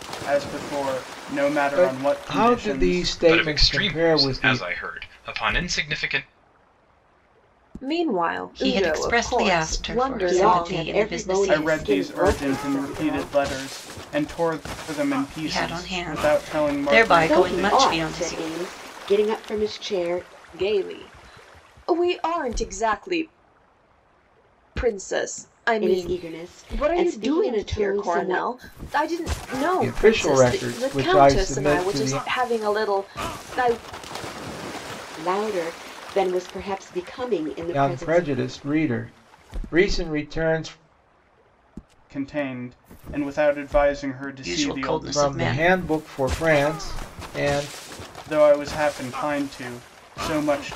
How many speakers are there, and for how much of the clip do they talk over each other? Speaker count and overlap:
six, about 35%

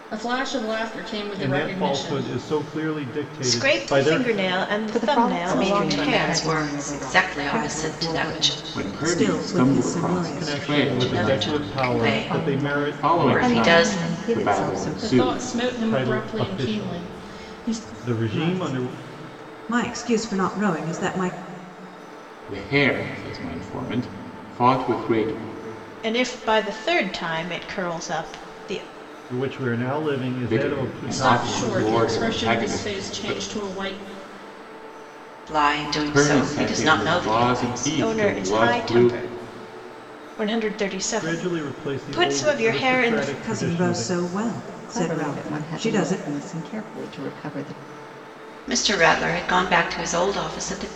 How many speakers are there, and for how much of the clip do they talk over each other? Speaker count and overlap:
seven, about 50%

